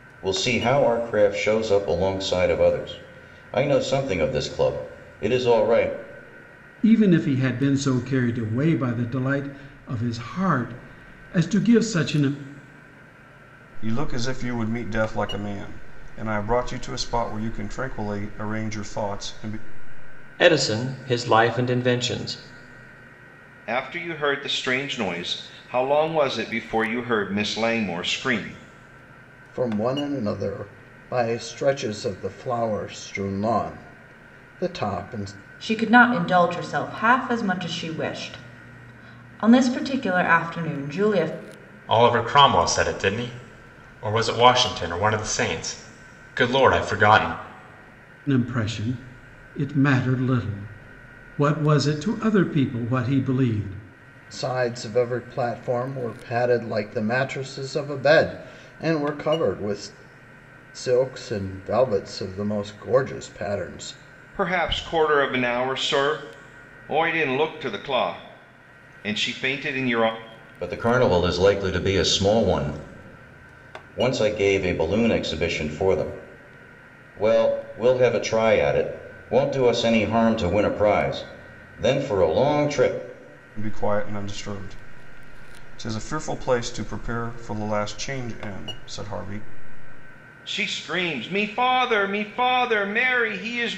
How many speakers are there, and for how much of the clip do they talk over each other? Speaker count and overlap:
eight, no overlap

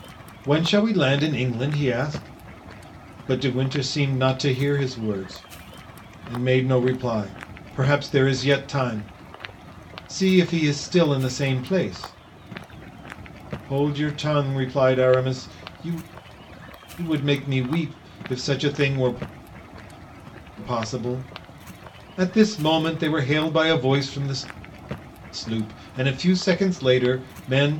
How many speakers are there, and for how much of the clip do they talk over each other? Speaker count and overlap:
one, no overlap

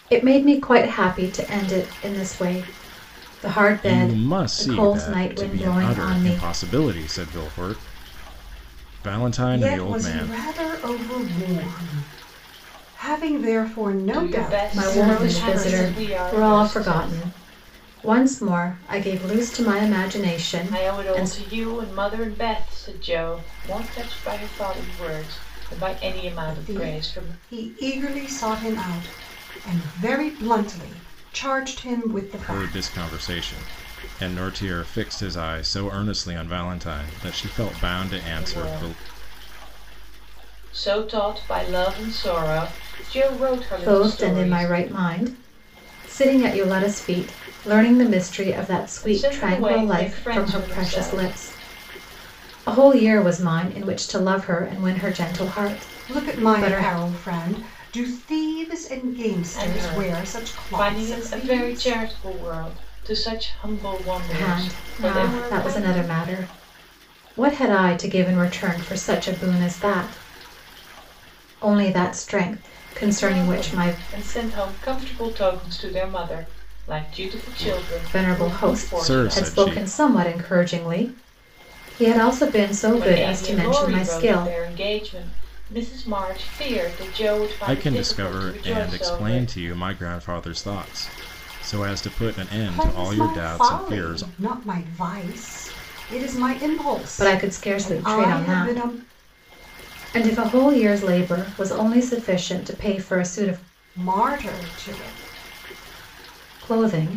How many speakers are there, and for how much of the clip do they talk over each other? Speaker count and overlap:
four, about 26%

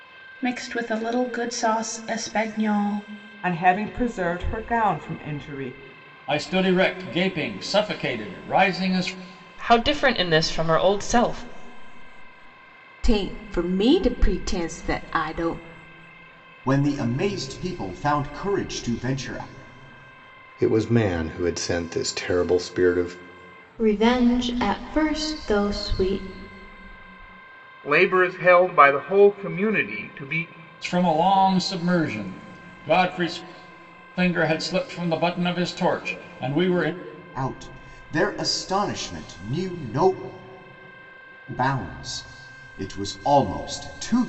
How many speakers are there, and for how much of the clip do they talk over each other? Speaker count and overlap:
nine, no overlap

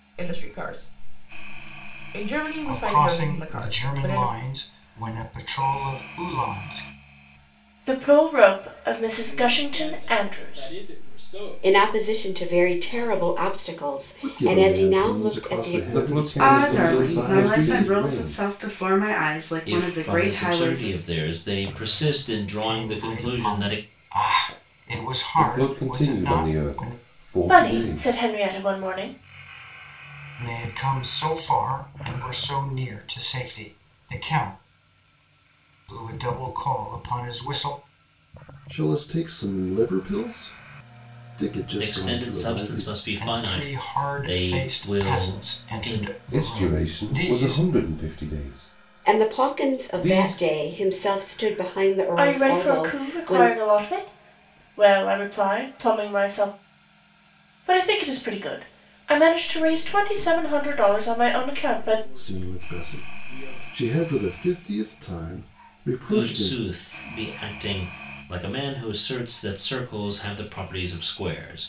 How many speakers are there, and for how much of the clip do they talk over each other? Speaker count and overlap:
nine, about 38%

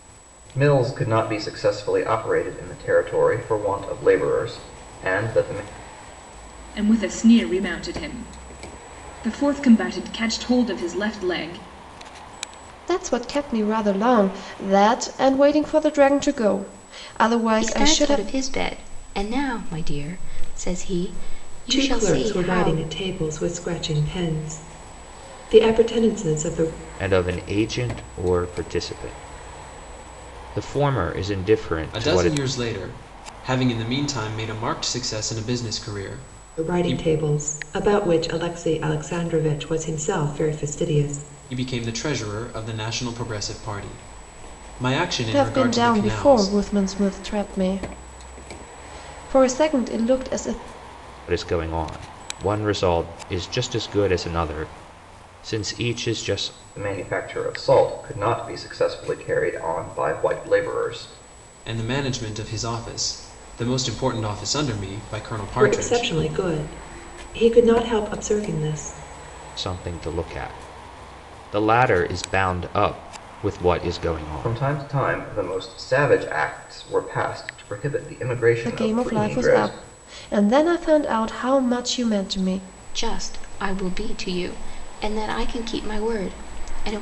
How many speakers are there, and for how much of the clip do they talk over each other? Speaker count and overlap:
seven, about 7%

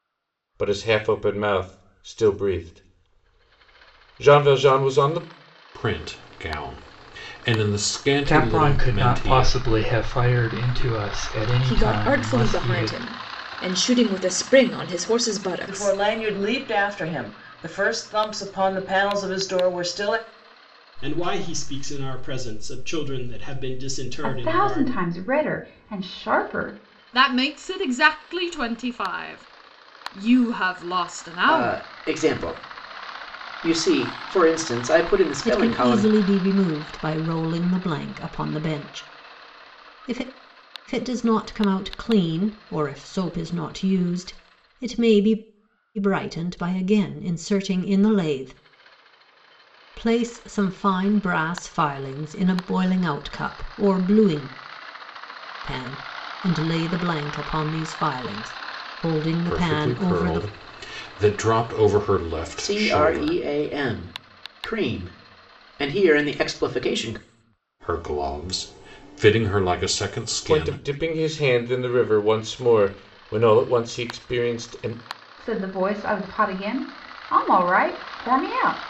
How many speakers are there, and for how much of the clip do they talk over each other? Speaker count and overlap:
ten, about 9%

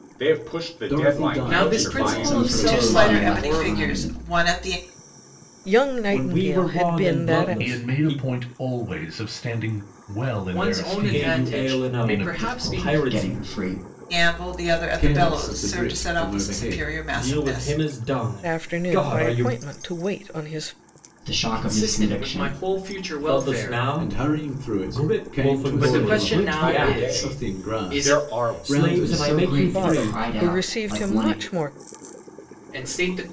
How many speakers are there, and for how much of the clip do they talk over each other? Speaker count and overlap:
eight, about 64%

